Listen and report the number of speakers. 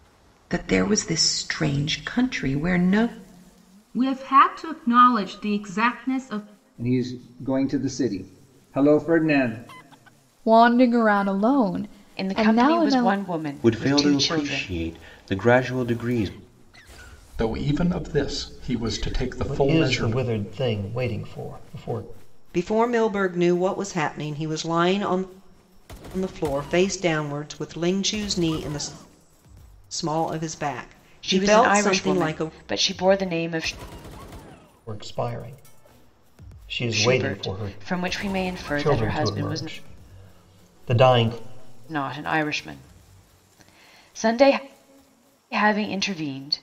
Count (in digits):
9